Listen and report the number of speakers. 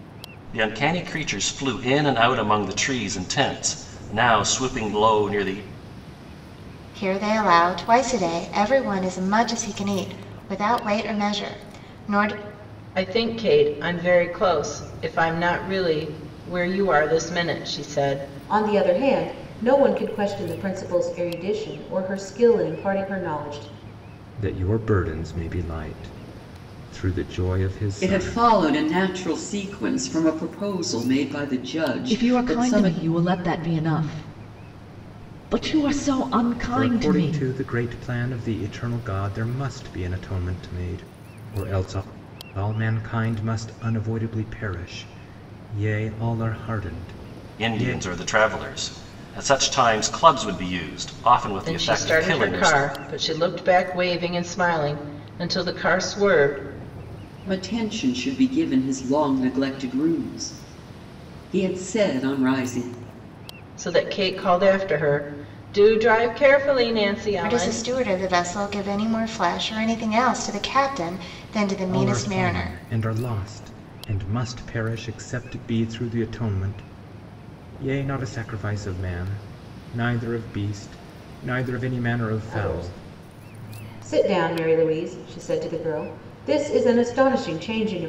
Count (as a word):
seven